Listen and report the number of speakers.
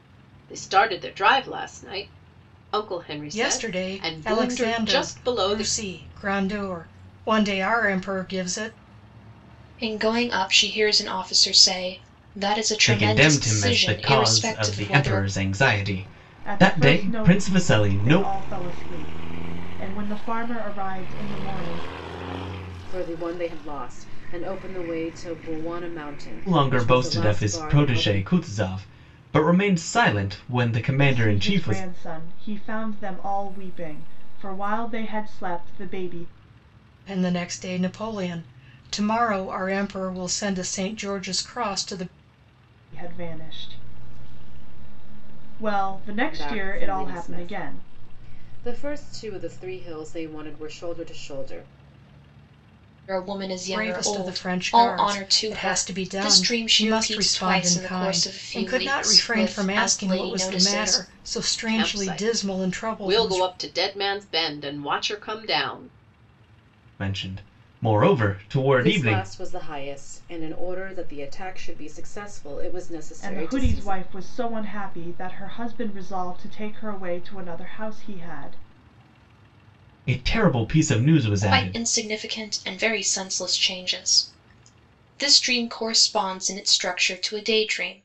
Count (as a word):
six